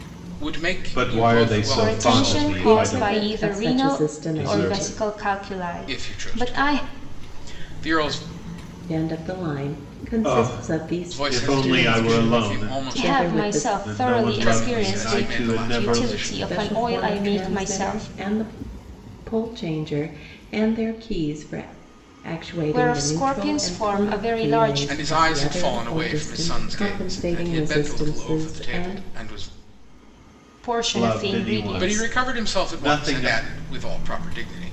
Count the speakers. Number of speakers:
4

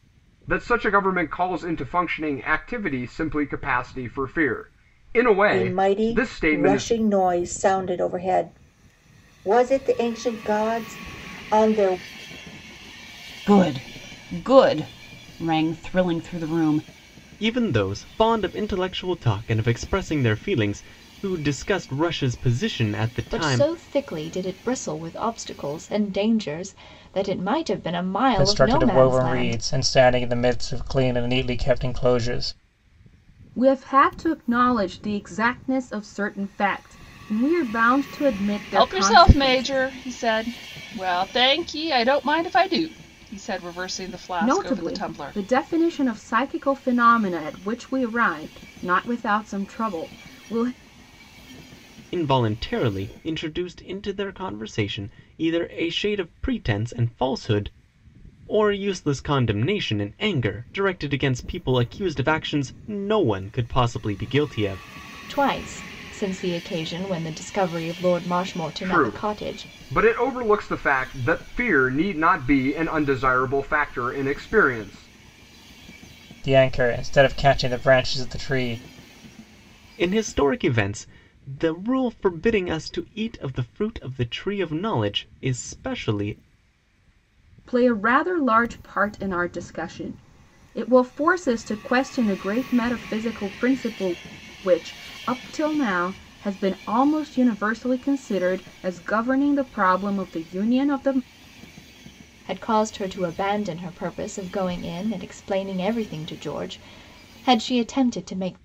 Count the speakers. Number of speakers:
8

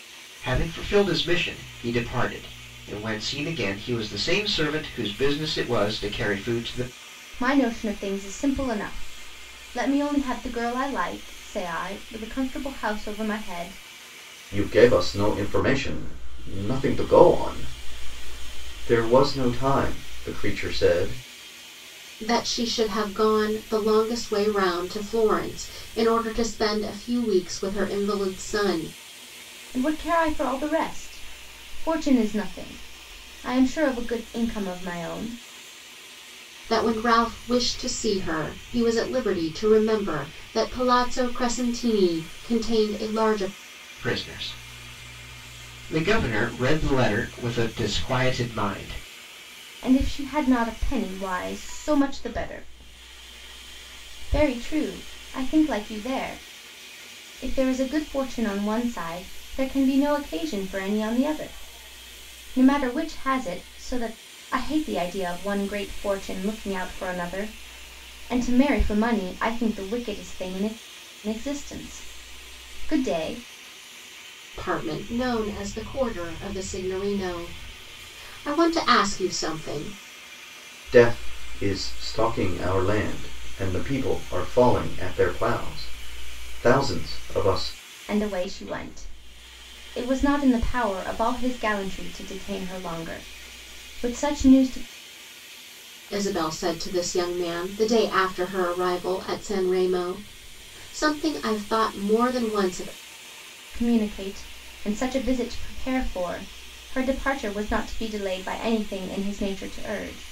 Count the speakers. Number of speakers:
4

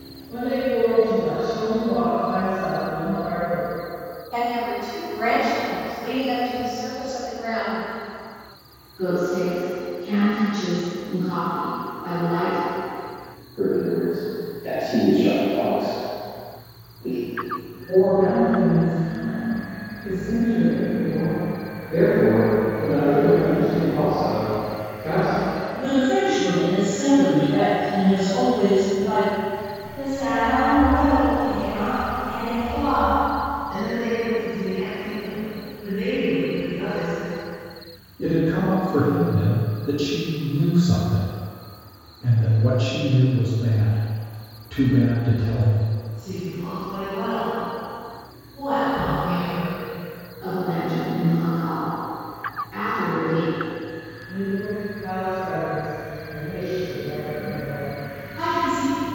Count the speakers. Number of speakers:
10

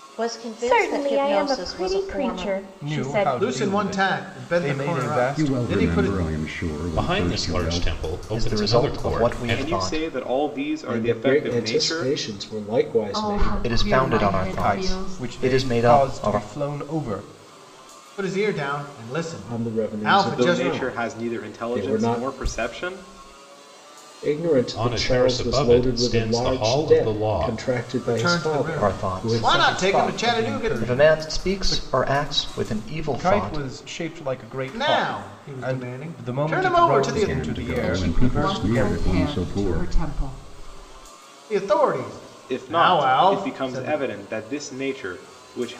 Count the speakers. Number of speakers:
10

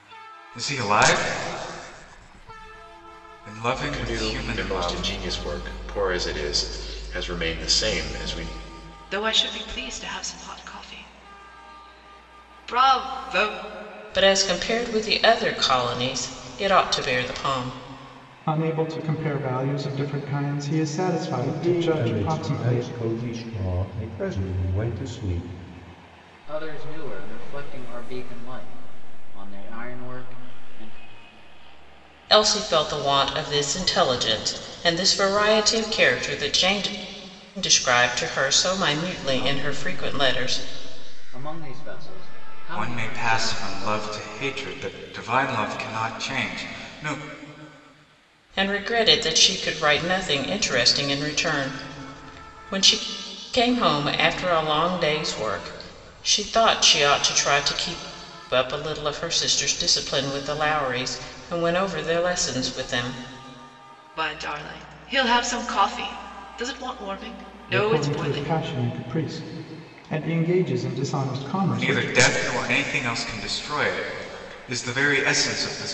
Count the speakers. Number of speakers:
7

